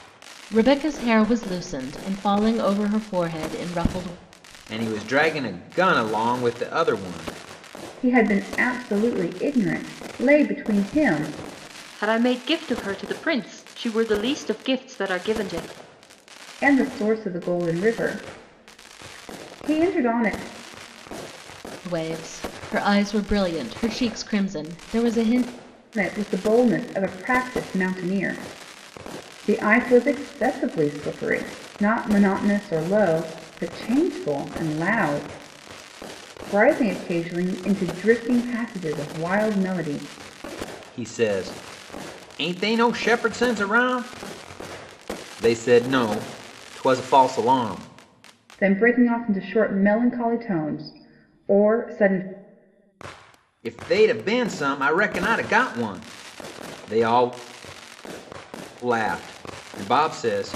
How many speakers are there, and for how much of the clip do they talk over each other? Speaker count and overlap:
4, no overlap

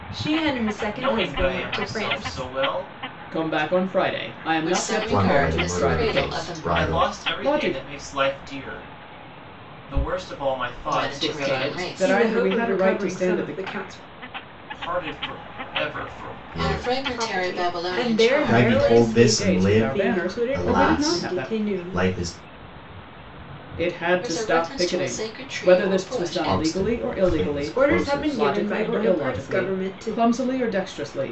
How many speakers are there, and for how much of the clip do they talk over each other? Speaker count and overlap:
5, about 61%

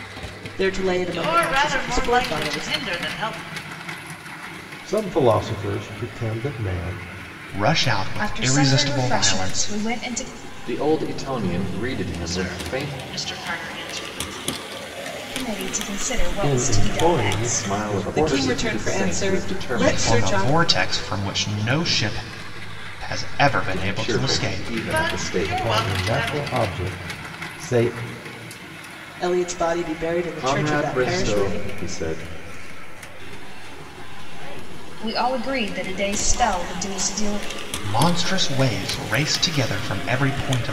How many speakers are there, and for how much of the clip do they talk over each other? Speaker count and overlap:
7, about 44%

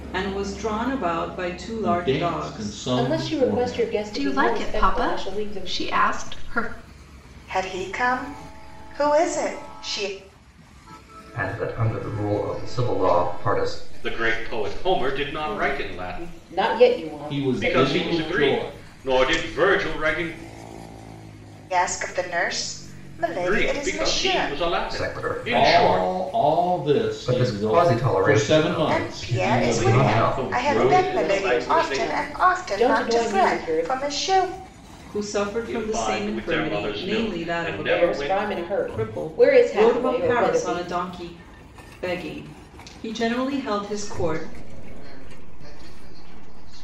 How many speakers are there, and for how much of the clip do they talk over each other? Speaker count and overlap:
8, about 52%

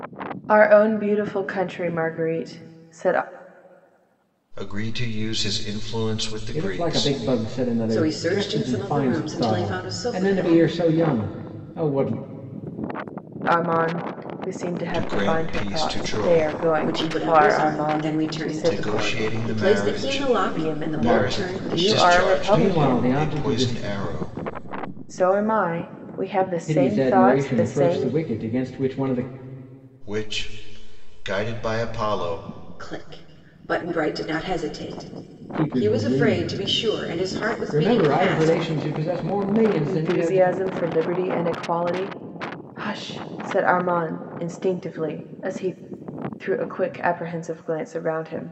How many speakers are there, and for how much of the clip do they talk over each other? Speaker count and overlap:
4, about 33%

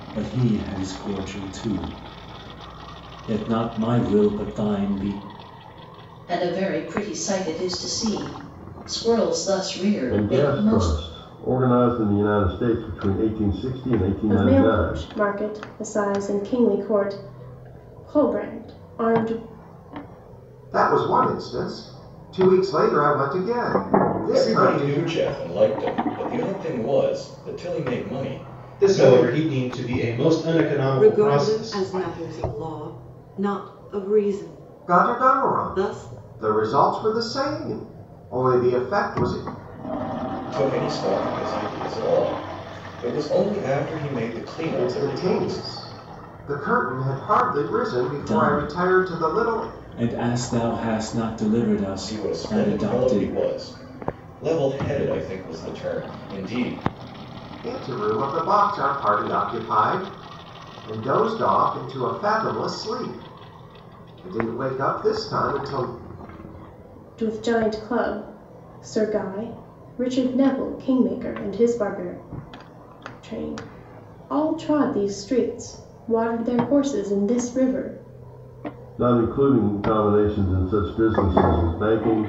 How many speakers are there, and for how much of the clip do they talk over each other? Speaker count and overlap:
8, about 11%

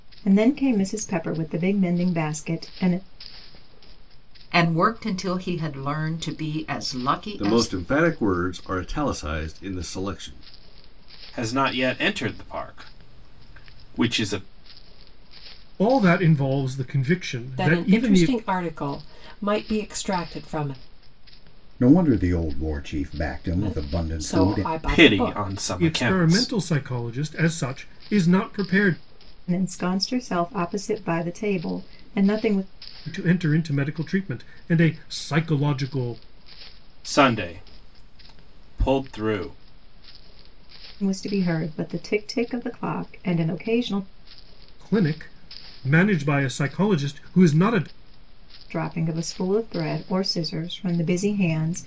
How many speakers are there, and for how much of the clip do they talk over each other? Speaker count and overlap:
7, about 7%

